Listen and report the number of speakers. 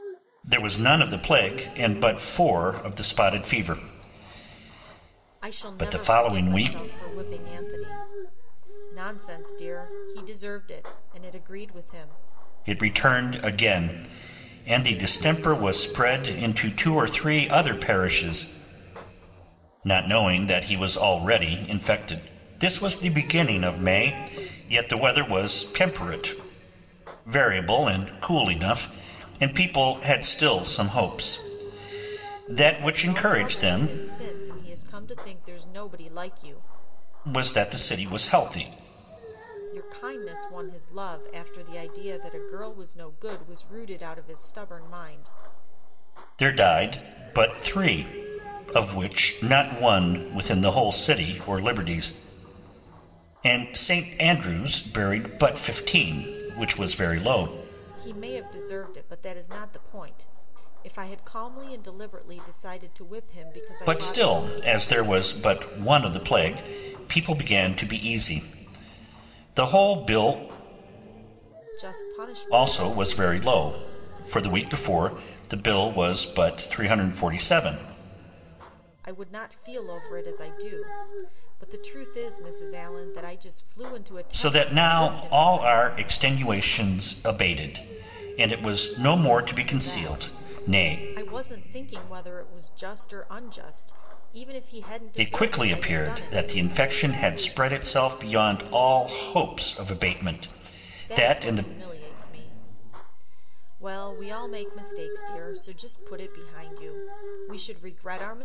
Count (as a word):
two